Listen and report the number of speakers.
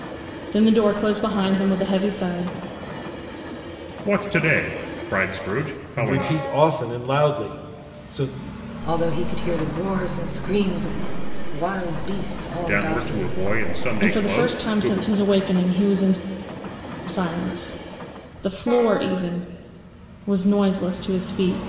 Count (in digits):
4